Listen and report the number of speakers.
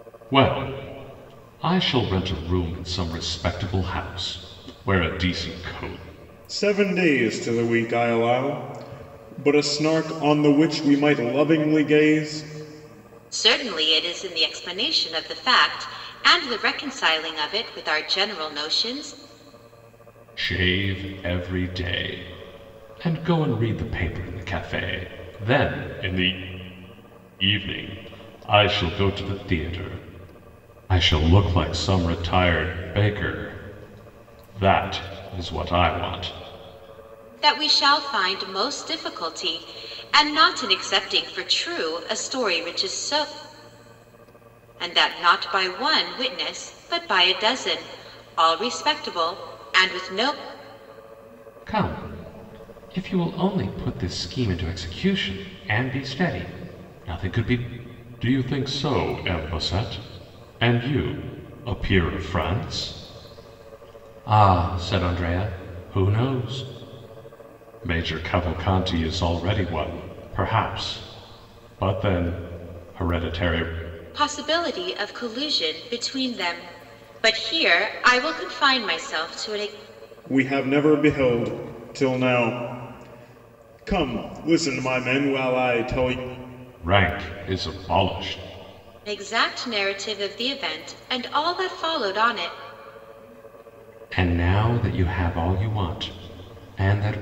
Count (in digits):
3